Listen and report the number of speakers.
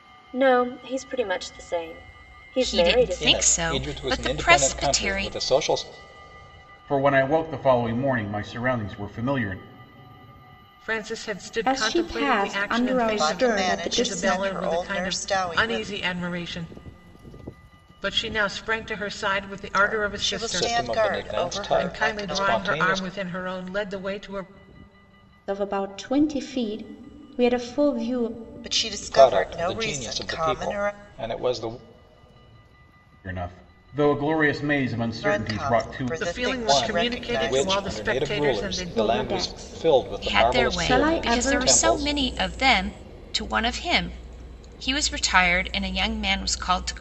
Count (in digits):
7